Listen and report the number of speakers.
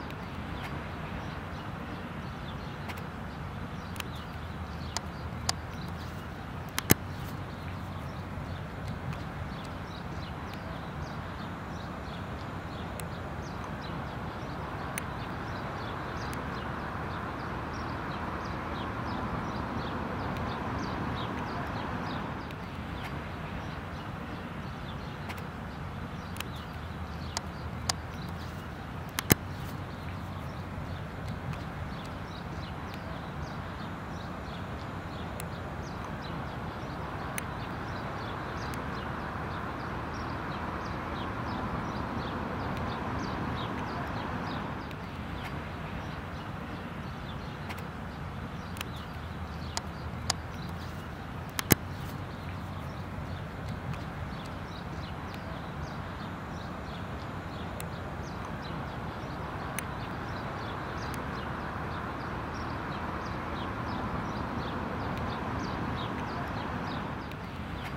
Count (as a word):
zero